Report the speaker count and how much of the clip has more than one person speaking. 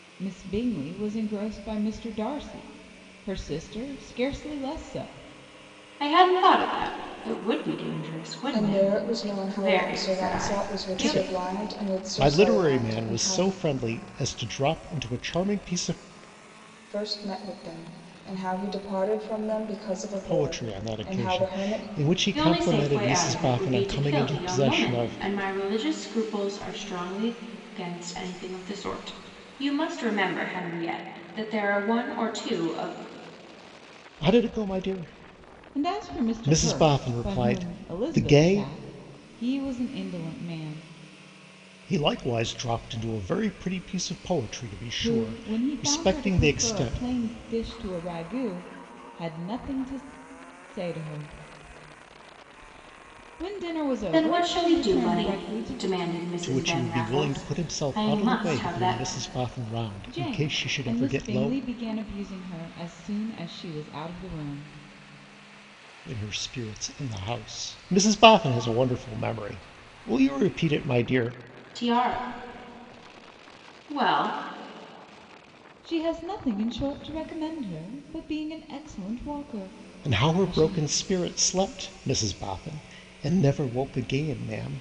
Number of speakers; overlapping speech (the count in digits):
4, about 26%